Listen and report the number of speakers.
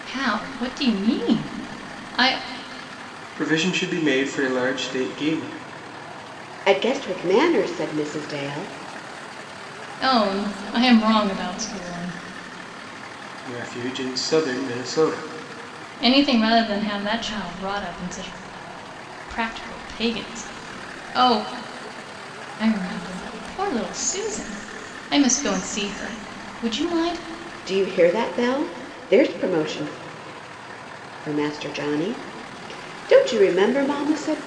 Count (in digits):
3